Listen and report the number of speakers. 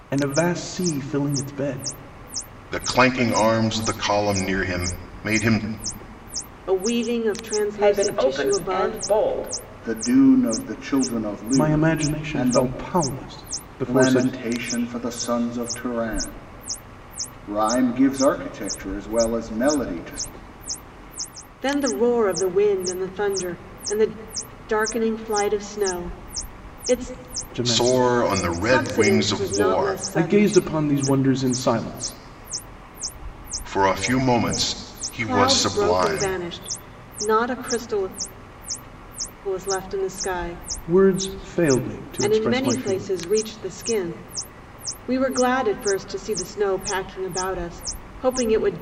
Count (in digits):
5